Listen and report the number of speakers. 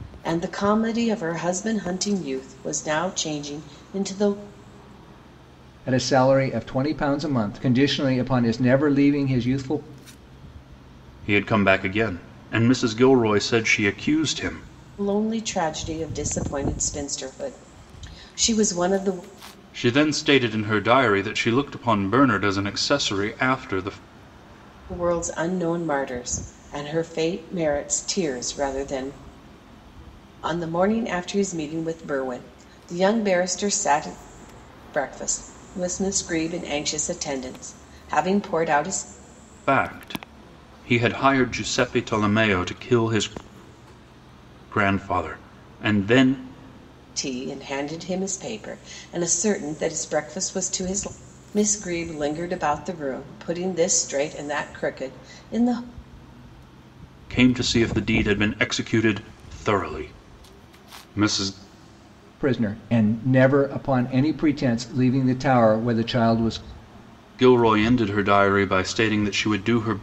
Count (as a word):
three